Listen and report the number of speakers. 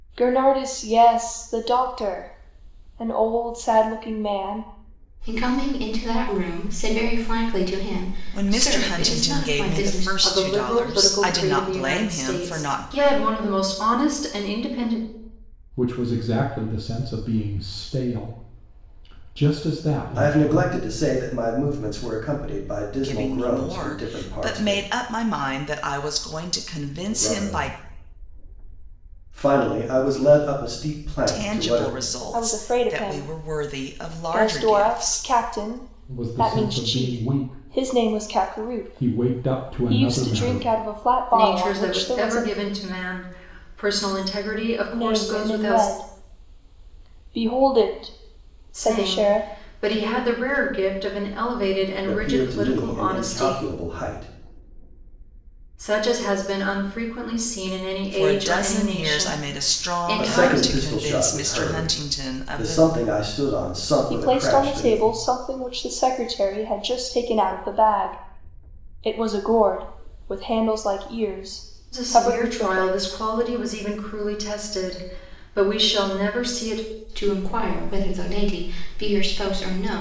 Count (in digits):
6